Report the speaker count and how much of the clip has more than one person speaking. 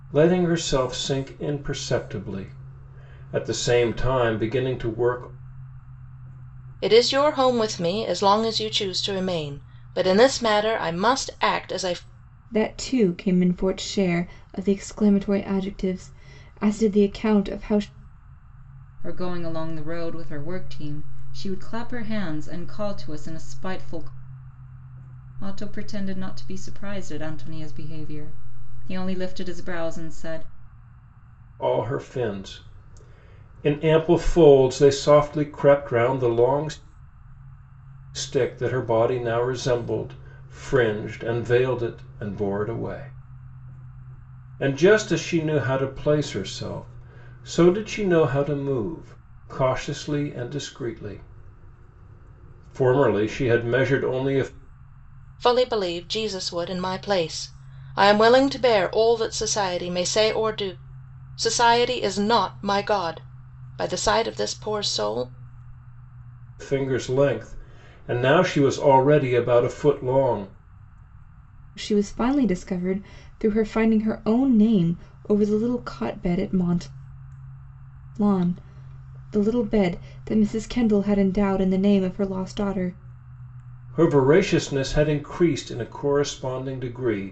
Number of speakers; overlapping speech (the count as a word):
four, no overlap